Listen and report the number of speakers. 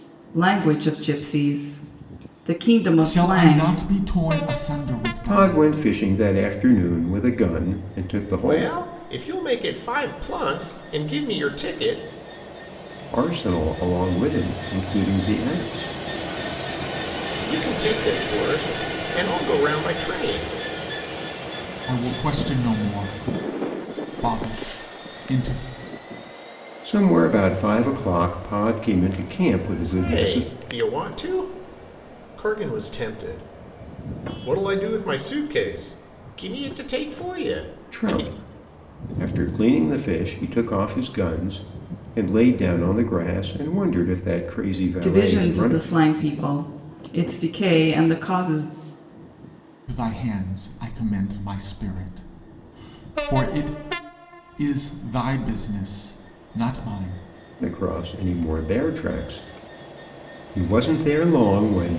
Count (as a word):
four